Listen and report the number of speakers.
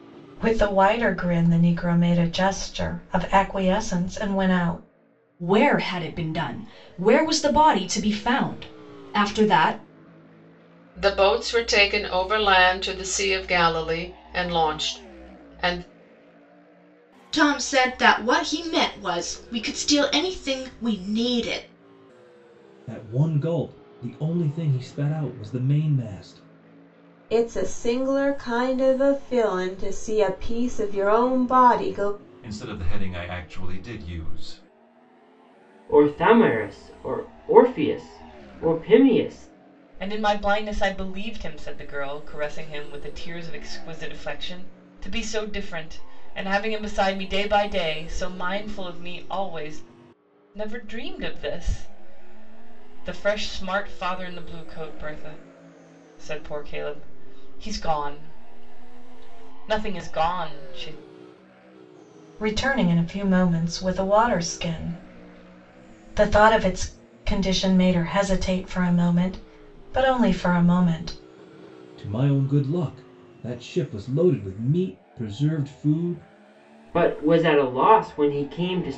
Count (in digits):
9